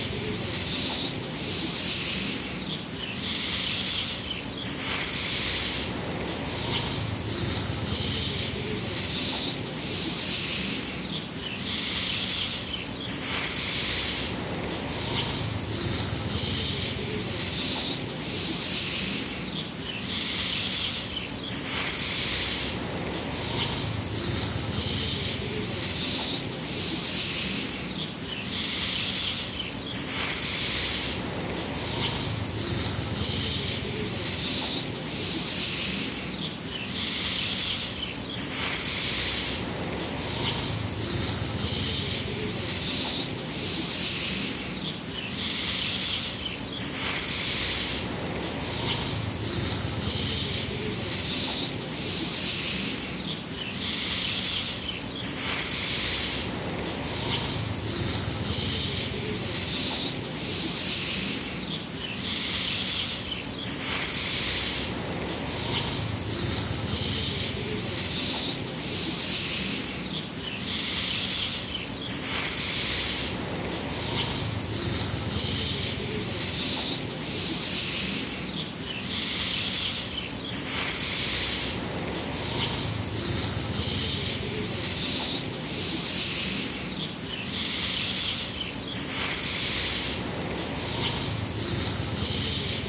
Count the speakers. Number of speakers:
zero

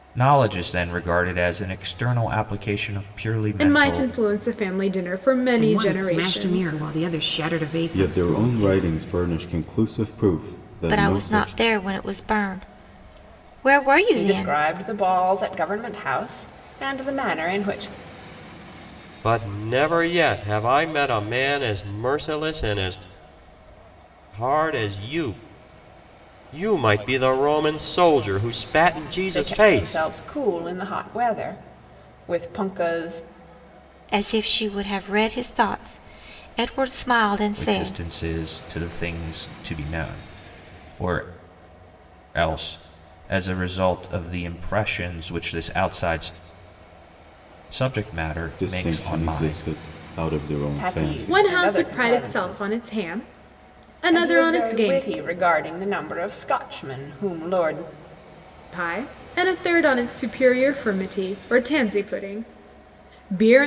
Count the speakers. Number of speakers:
seven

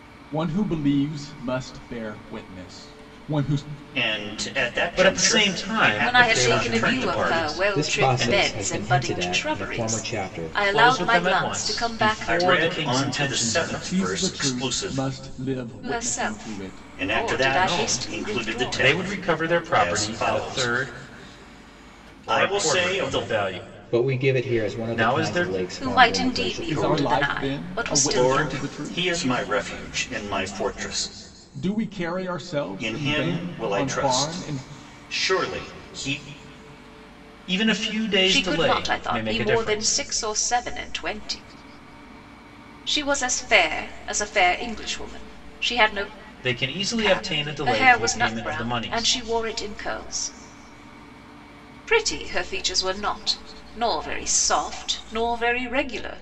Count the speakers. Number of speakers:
five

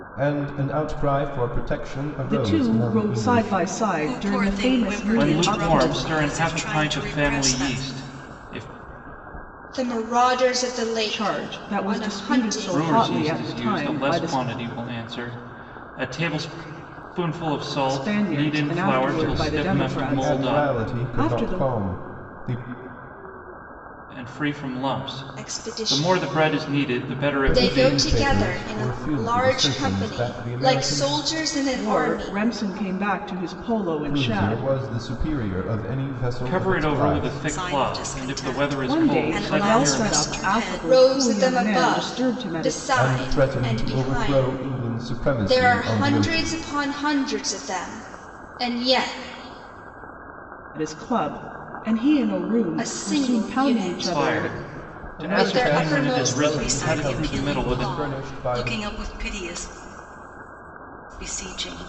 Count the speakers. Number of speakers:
five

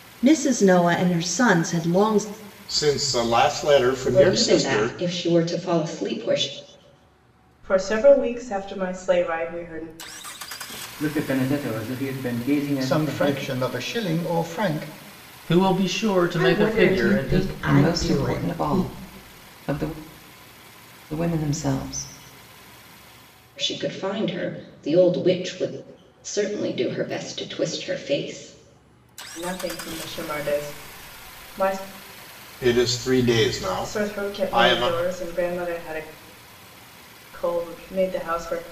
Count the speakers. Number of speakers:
nine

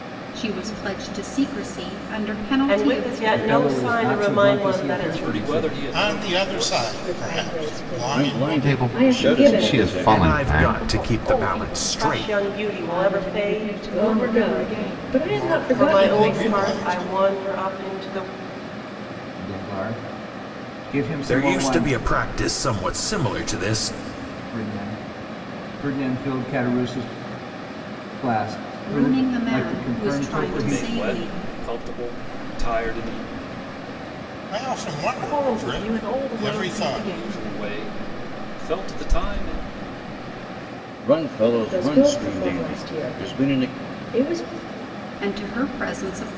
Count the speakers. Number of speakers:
ten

